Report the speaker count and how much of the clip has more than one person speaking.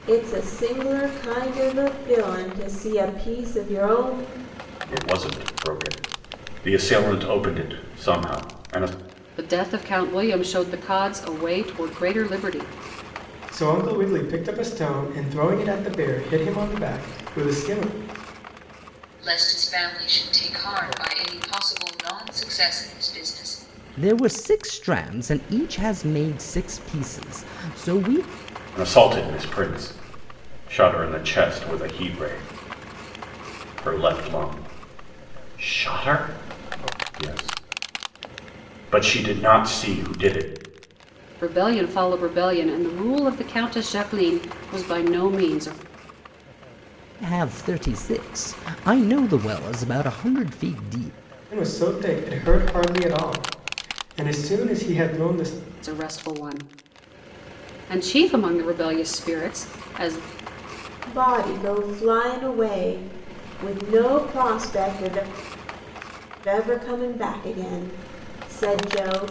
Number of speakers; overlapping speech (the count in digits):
6, no overlap